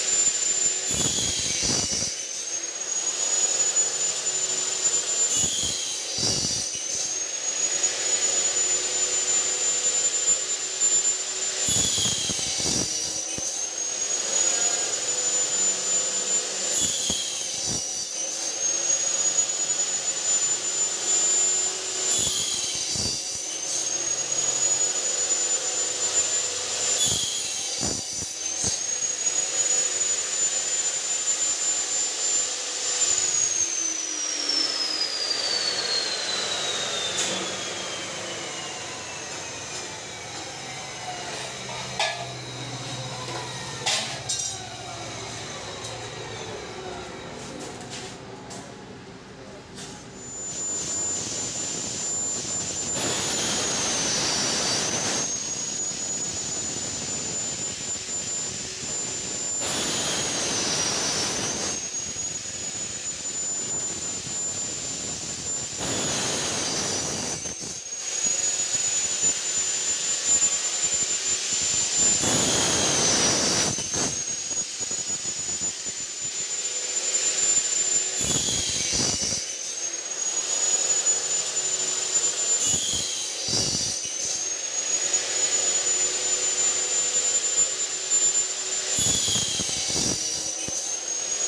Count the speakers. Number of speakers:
0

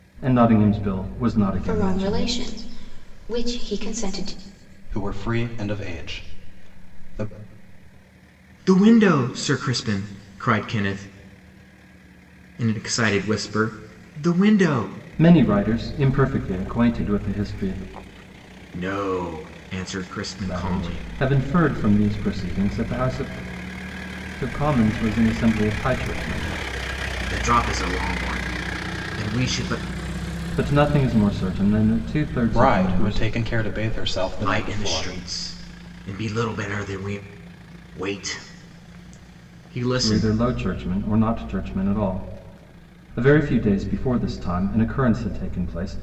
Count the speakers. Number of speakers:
4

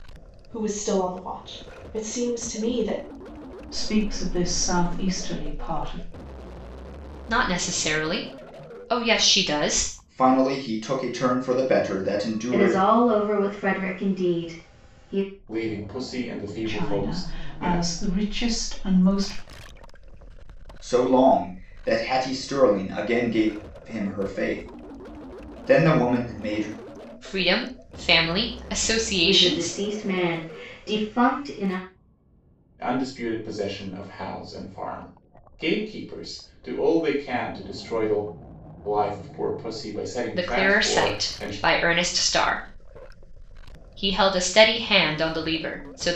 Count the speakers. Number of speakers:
6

